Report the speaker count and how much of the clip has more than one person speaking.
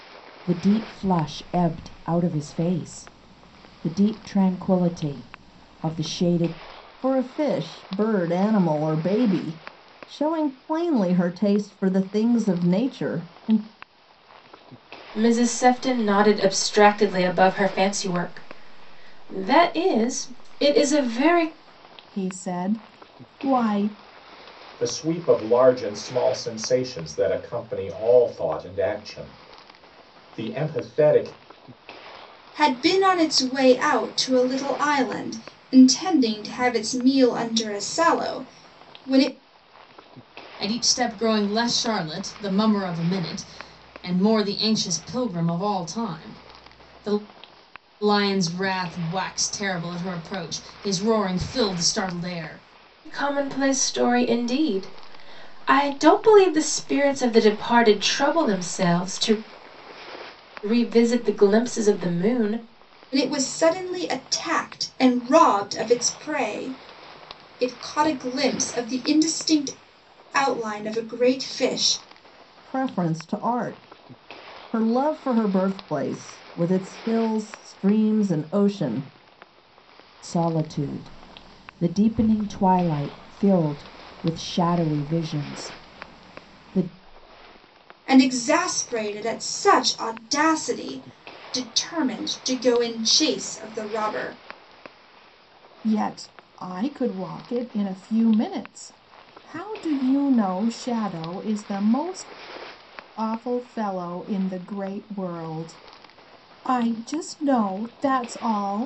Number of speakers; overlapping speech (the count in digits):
7, no overlap